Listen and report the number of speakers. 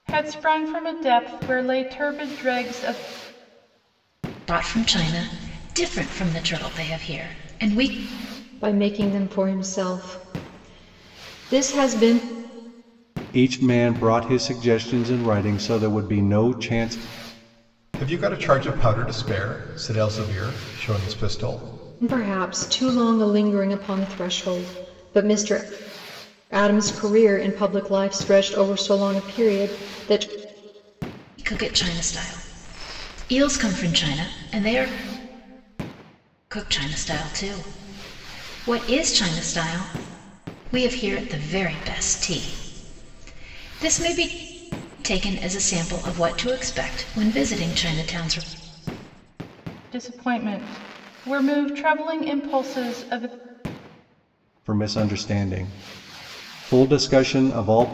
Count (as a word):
five